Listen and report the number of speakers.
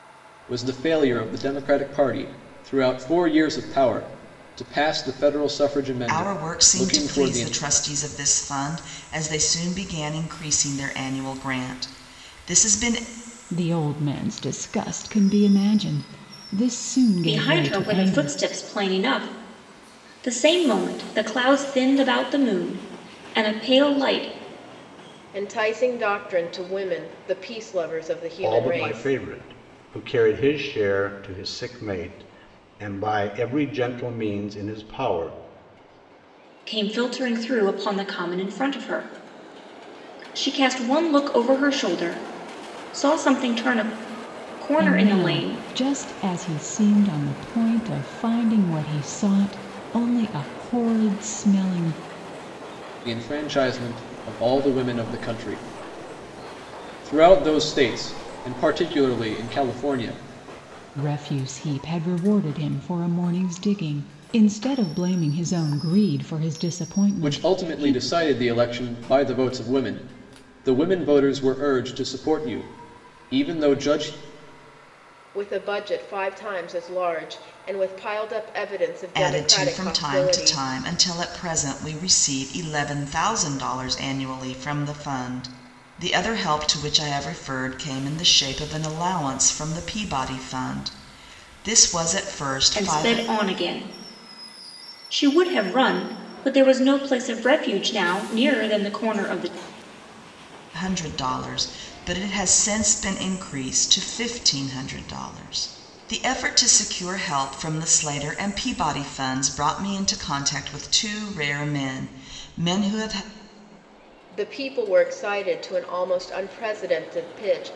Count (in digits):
6